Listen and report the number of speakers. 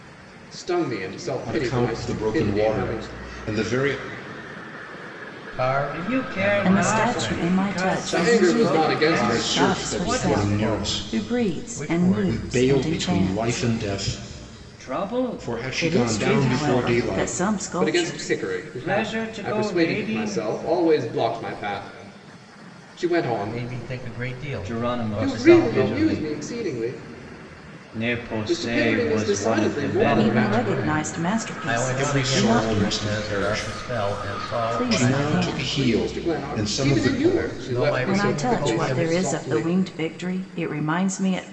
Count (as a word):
five